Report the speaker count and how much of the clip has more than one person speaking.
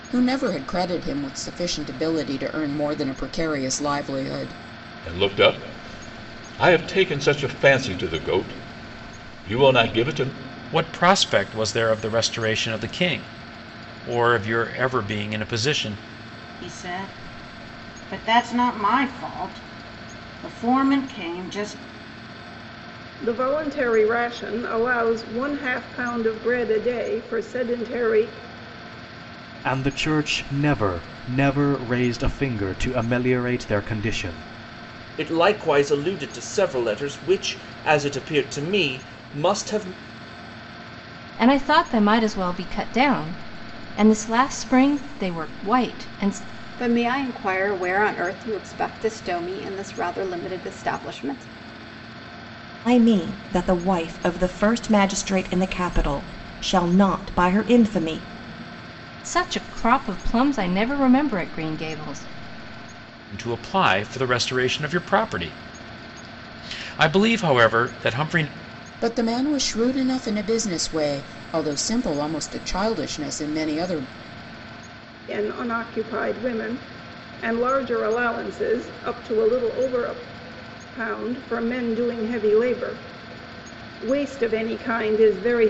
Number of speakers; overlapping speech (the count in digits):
10, no overlap